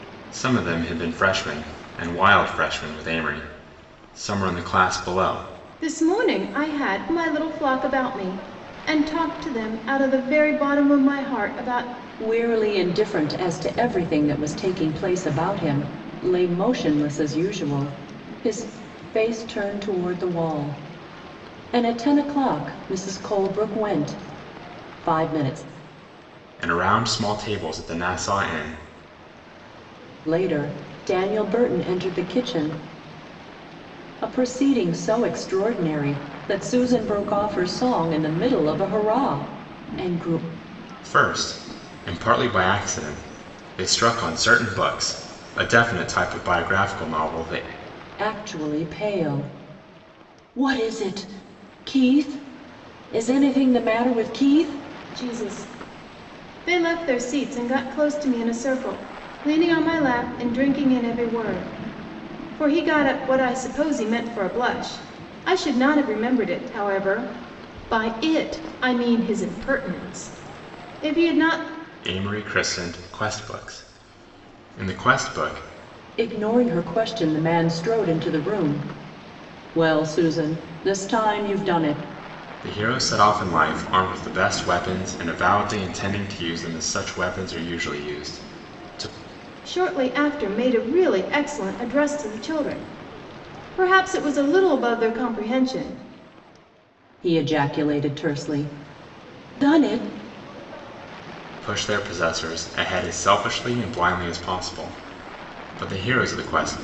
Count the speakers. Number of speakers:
3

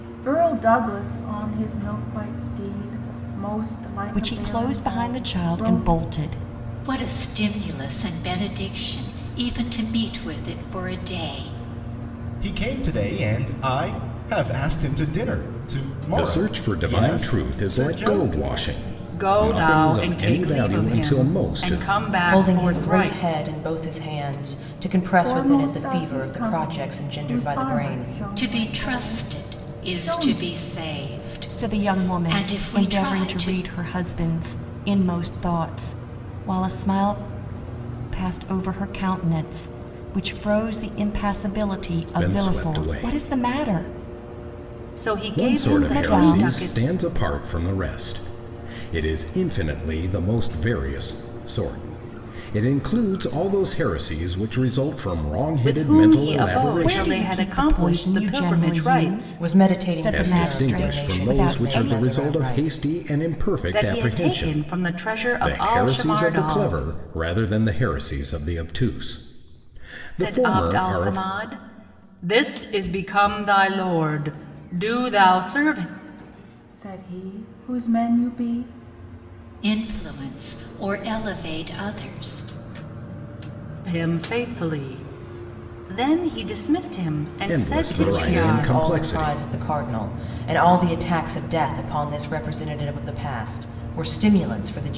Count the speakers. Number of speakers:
7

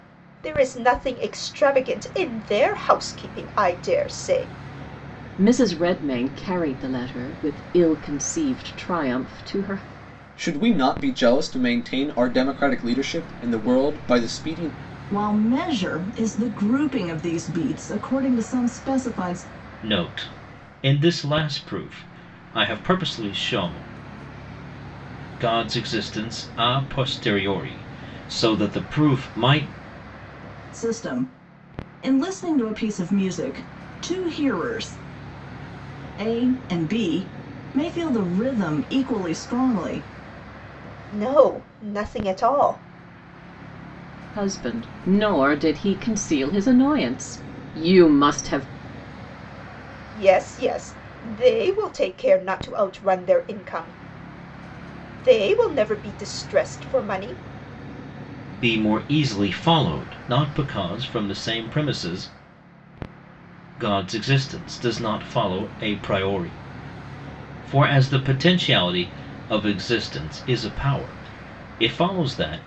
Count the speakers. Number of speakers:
5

